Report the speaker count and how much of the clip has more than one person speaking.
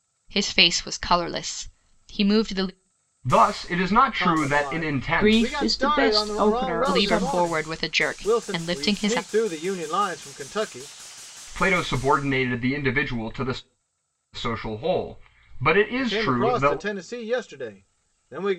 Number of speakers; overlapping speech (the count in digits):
4, about 33%